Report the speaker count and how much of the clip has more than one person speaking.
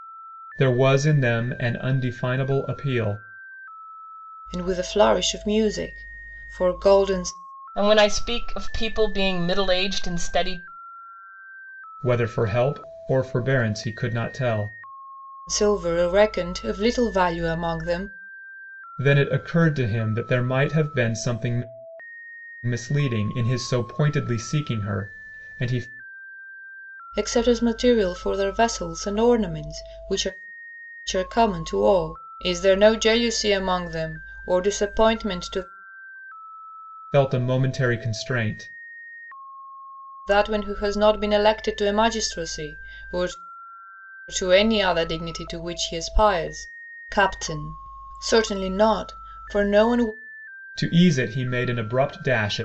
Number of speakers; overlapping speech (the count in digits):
3, no overlap